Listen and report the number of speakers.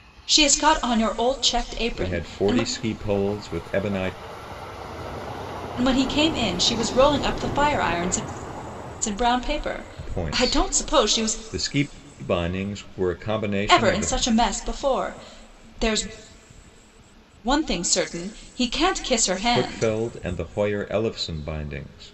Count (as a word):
two